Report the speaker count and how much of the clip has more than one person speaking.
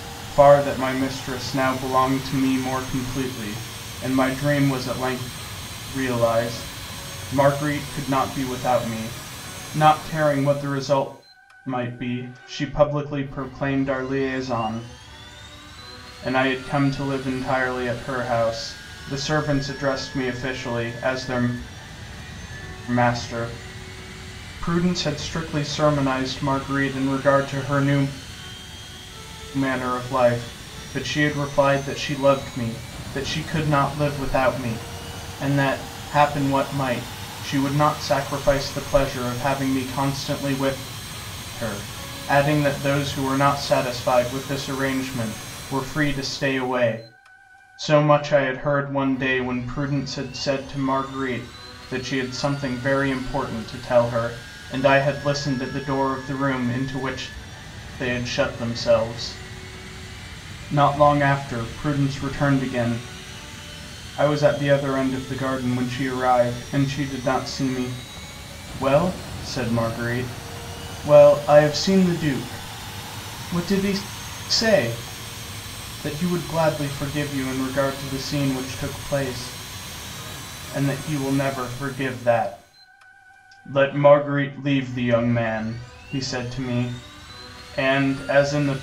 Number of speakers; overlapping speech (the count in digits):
1, no overlap